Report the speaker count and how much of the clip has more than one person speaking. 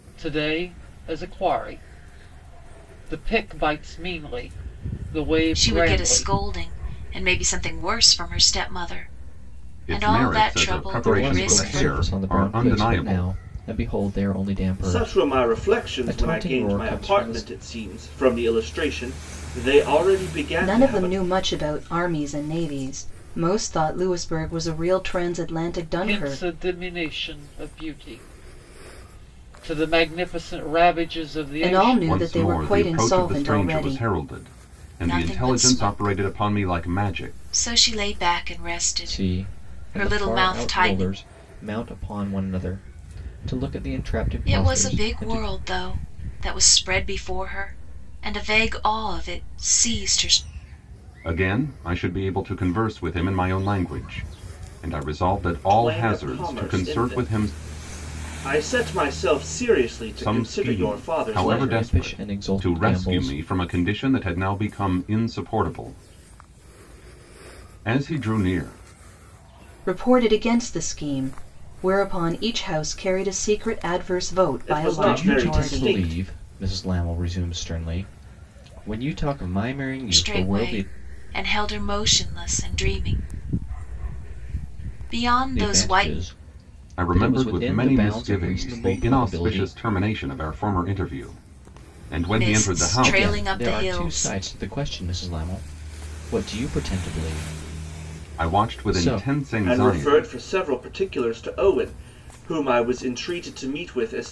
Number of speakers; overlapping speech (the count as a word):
six, about 29%